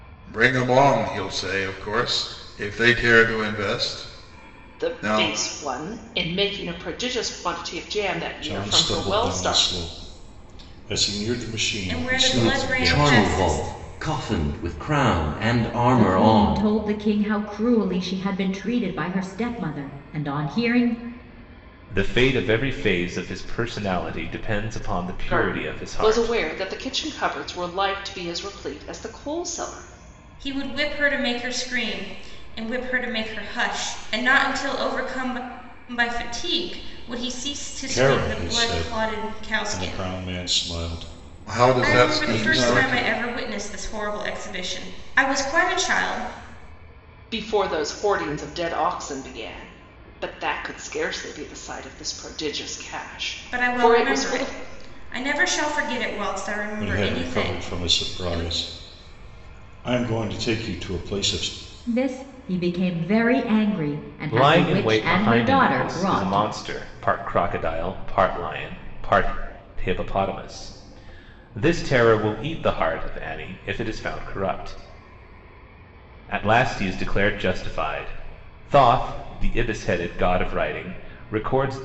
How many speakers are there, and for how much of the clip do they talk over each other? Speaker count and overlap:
7, about 18%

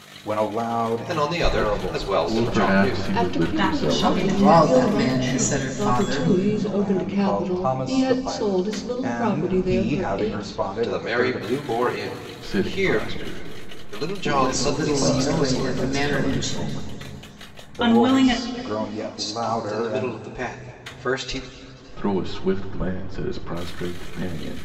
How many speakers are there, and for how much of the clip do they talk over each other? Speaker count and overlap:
6, about 61%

